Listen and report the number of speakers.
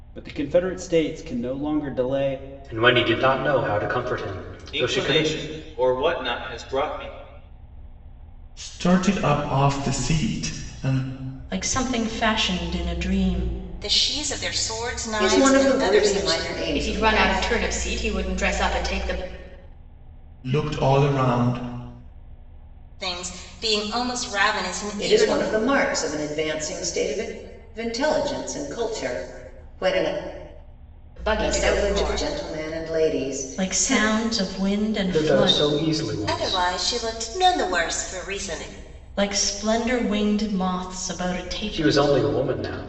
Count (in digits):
8